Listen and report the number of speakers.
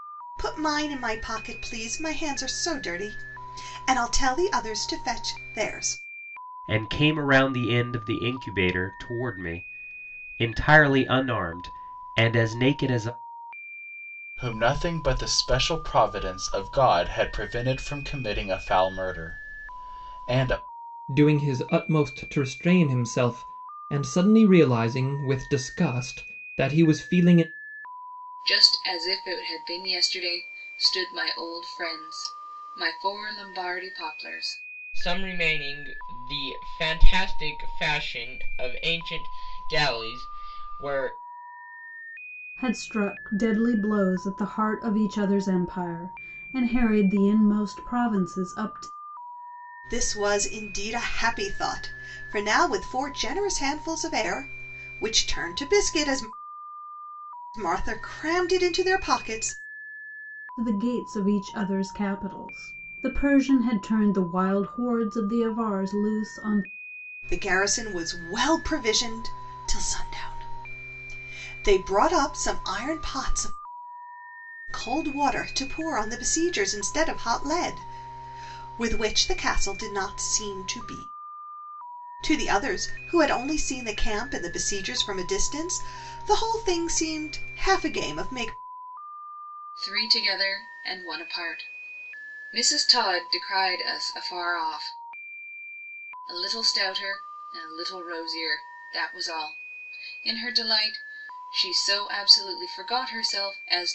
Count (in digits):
7